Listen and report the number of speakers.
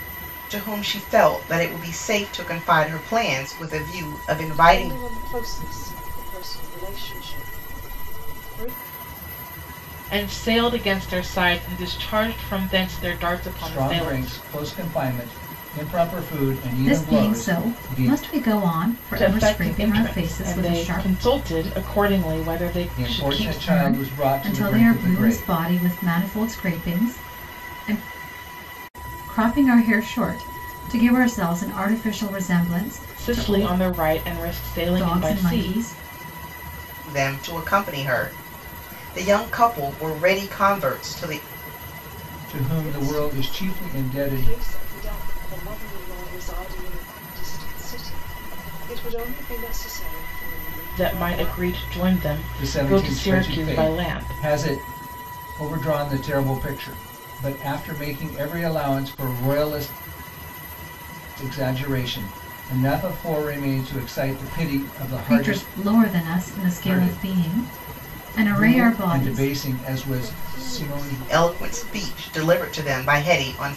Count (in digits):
5